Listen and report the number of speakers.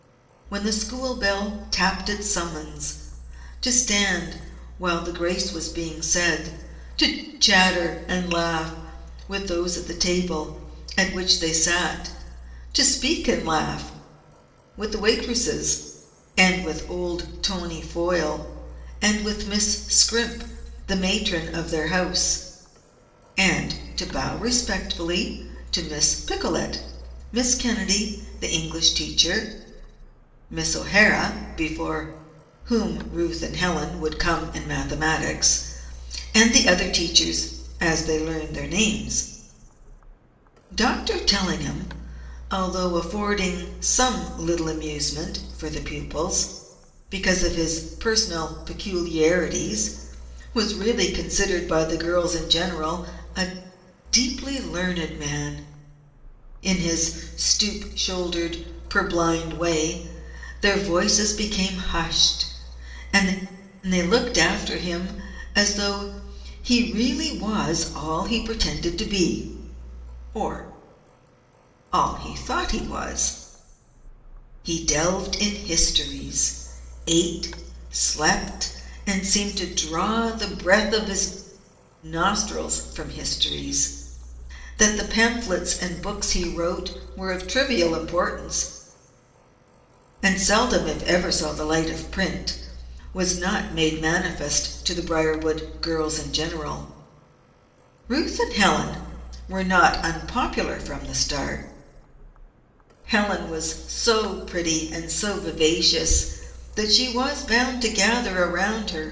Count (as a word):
one